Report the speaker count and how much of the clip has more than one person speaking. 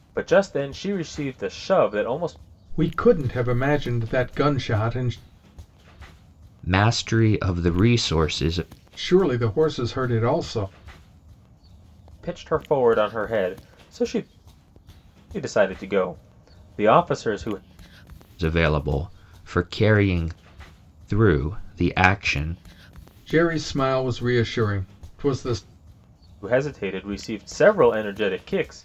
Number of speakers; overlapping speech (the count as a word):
three, no overlap